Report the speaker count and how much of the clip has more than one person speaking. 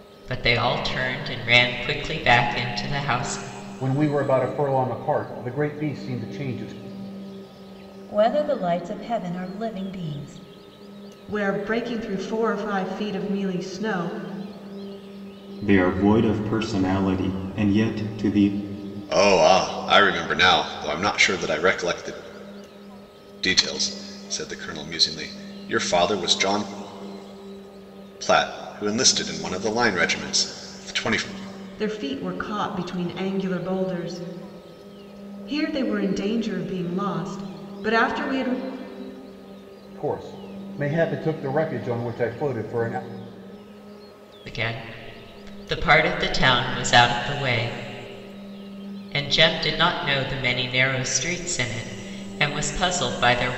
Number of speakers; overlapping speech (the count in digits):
6, no overlap